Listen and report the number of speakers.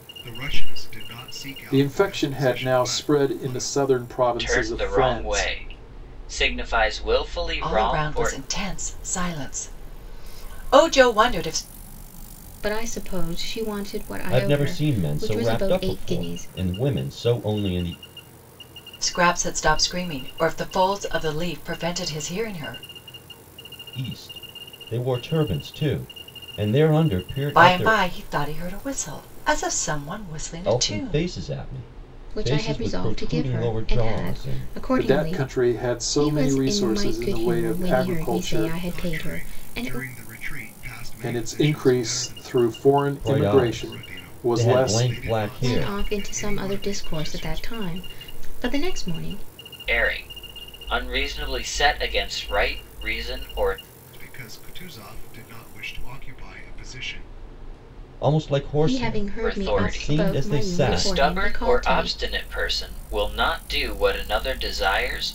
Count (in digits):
6